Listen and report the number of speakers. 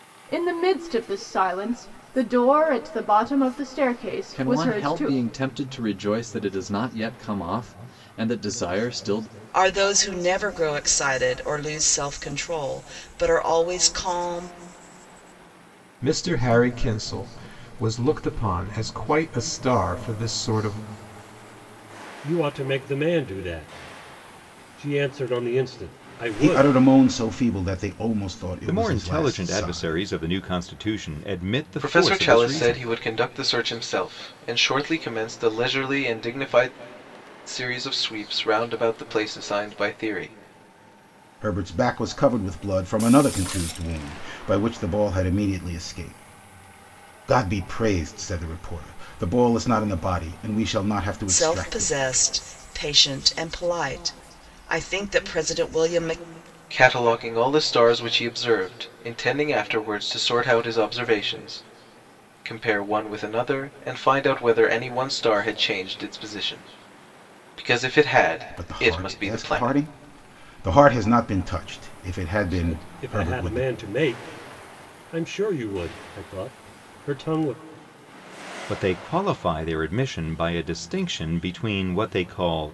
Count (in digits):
8